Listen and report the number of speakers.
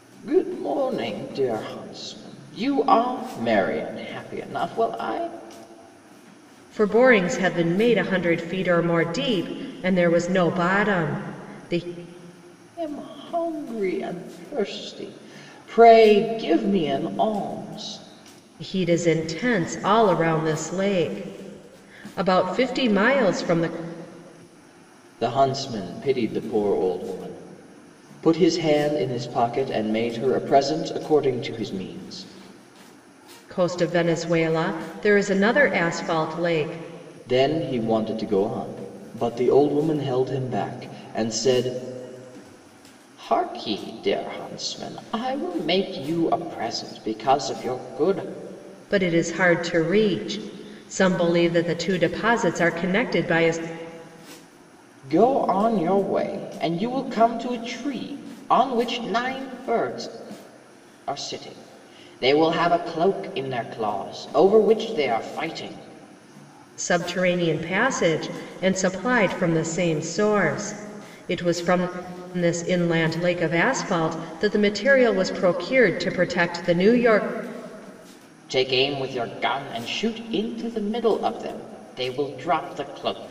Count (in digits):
2